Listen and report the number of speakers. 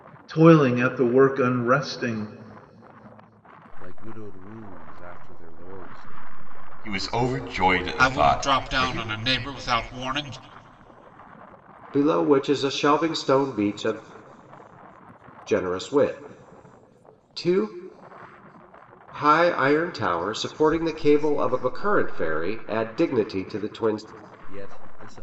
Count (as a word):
five